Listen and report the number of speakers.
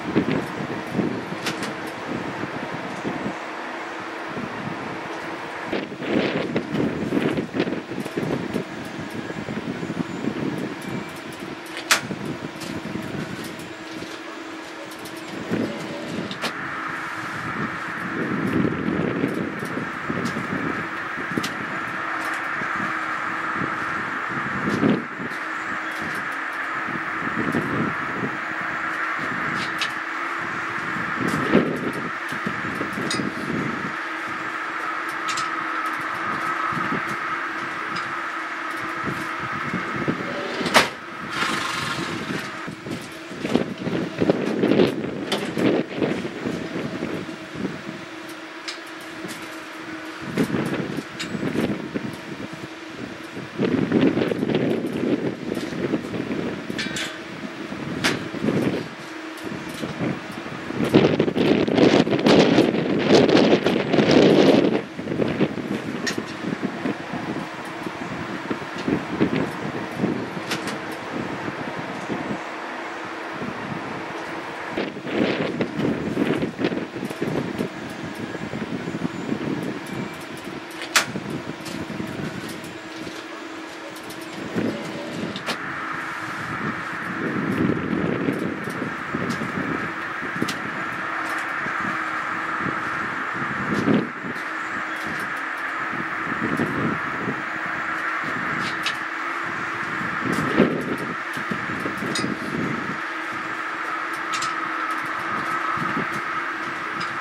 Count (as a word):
zero